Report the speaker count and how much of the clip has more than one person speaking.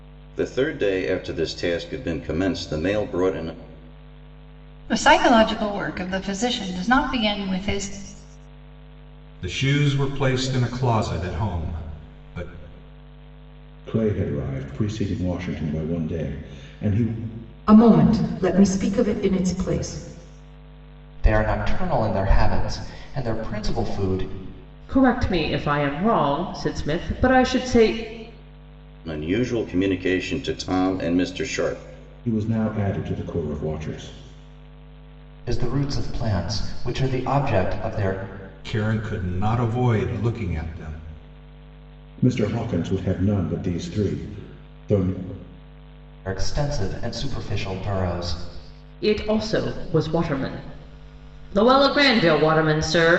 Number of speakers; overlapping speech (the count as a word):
seven, no overlap